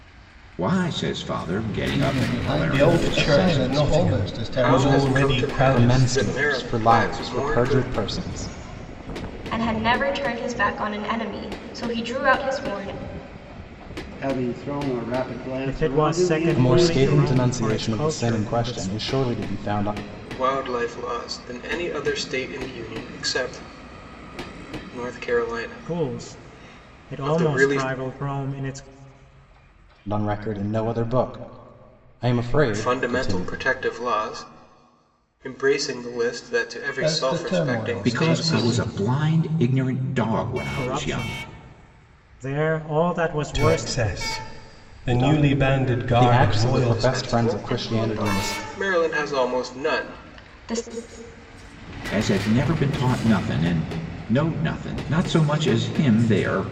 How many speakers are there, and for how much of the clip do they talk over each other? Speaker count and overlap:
8, about 37%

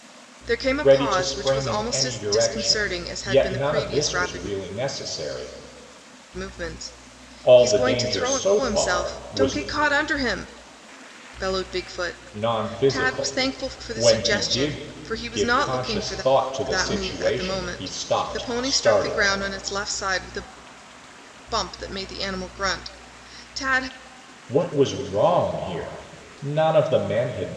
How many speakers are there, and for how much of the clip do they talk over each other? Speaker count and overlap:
2, about 41%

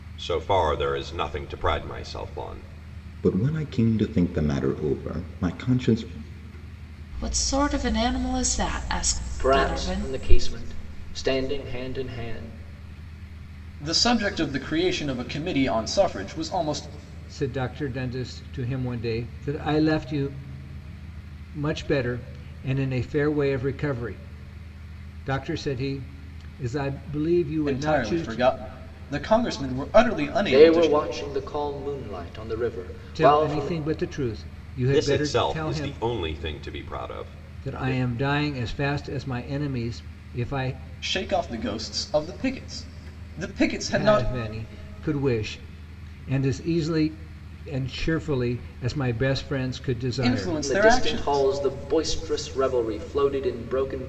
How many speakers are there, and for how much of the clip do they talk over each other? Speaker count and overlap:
6, about 11%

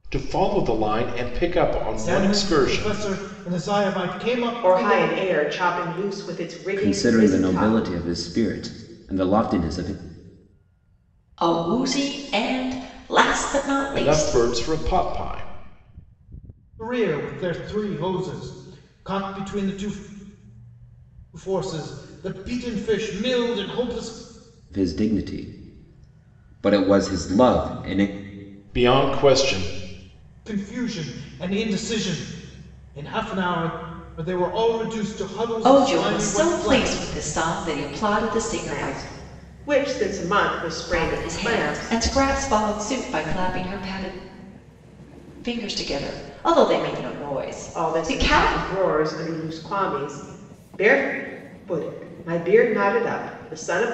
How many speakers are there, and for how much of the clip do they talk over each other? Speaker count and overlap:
5, about 13%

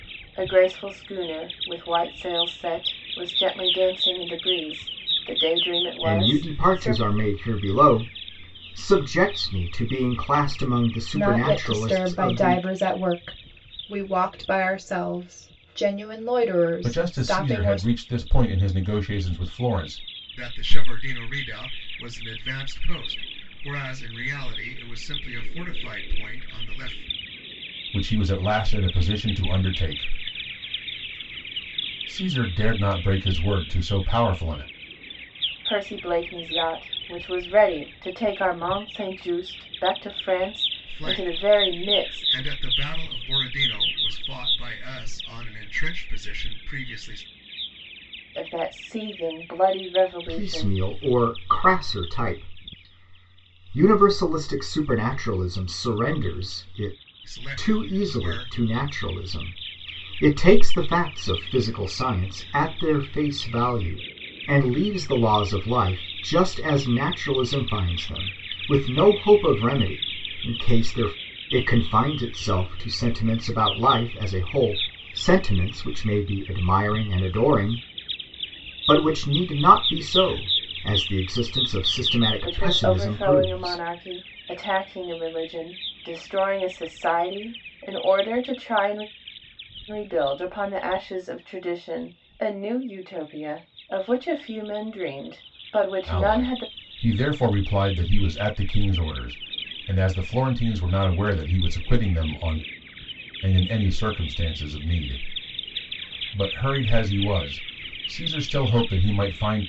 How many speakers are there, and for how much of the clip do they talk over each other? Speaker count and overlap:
5, about 8%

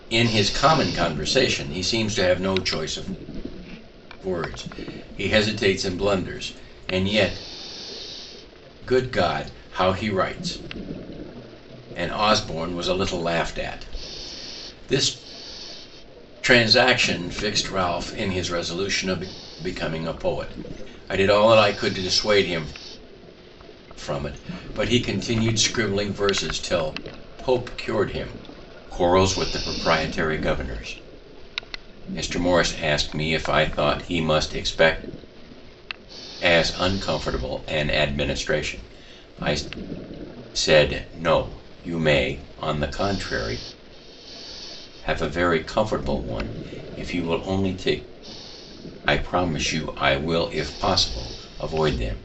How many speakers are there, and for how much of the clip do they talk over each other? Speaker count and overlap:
1, no overlap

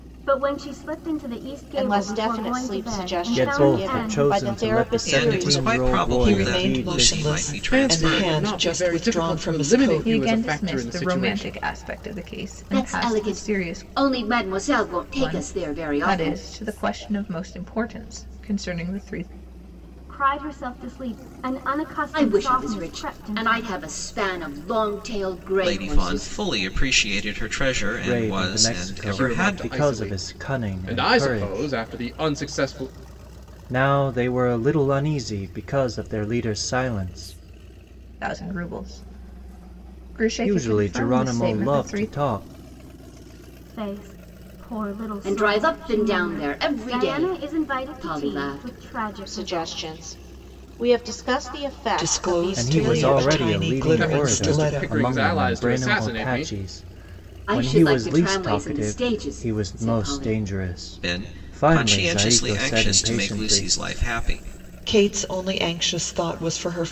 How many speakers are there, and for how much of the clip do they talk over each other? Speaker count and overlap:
8, about 52%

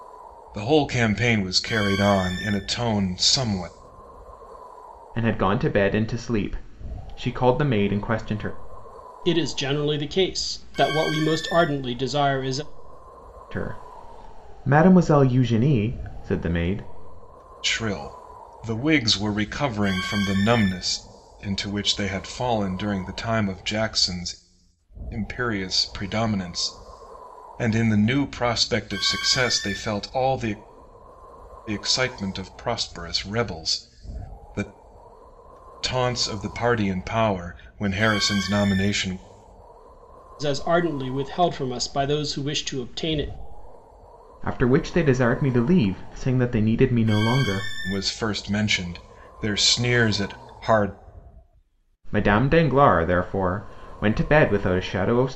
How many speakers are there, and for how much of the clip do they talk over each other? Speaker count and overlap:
3, no overlap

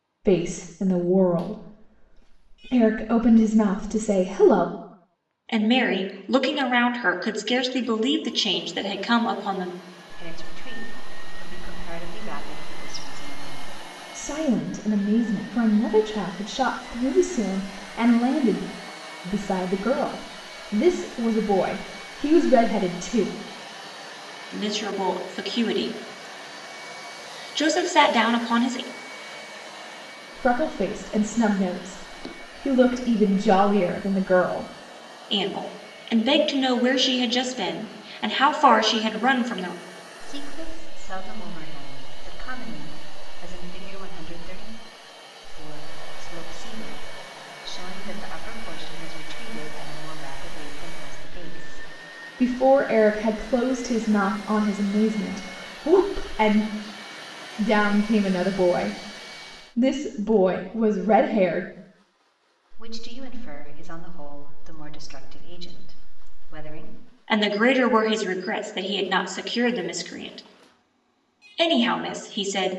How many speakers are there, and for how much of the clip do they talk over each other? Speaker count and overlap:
3, no overlap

